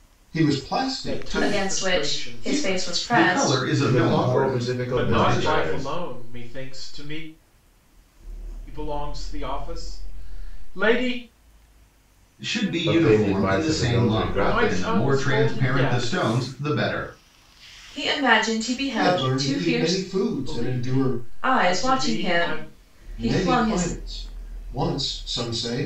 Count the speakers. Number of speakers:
five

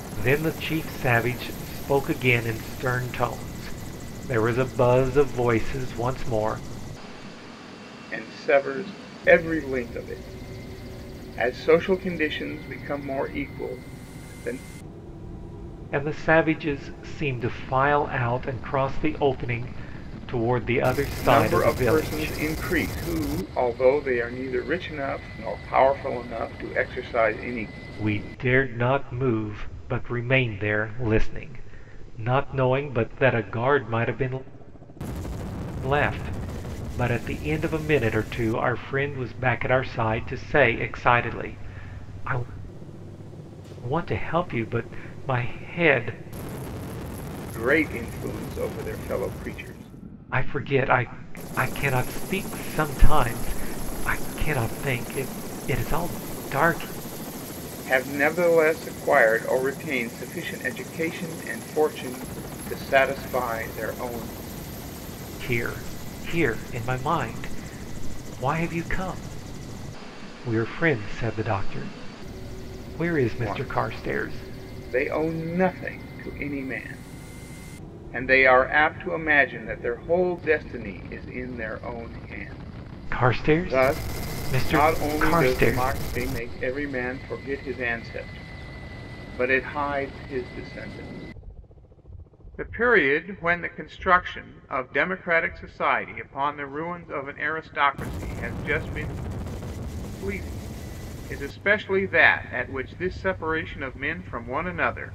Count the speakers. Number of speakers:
two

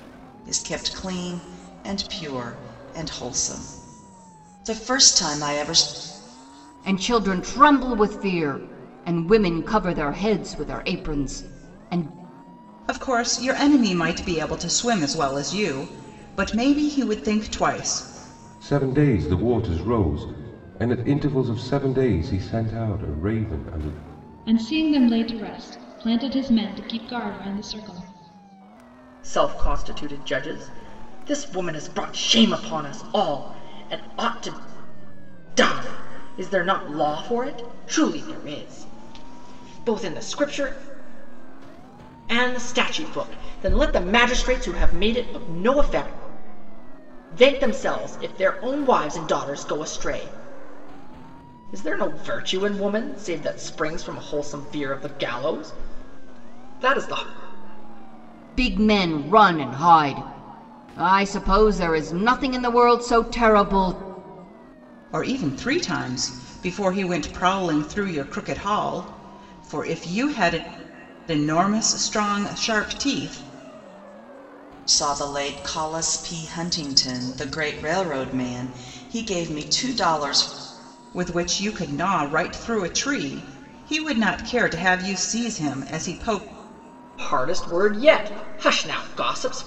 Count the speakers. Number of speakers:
six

